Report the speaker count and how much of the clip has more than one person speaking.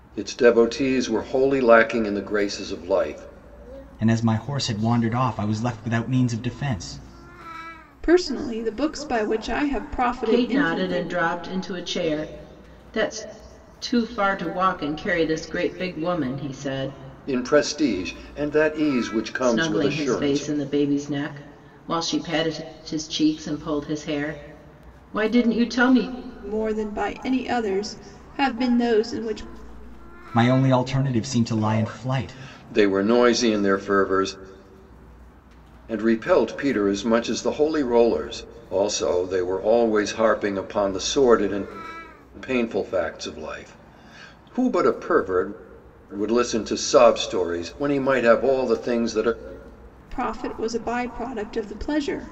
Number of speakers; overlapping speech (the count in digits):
4, about 6%